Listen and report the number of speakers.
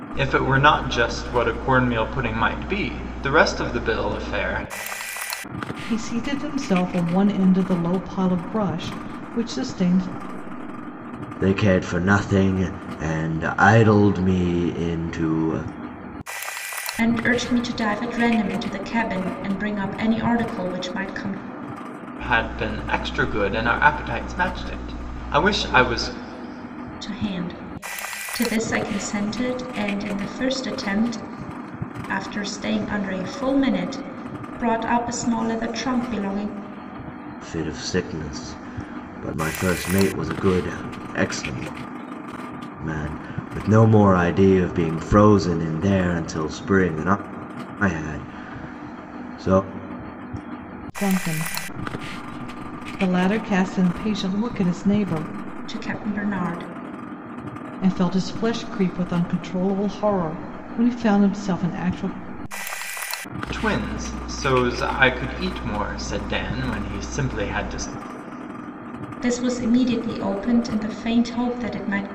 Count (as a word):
four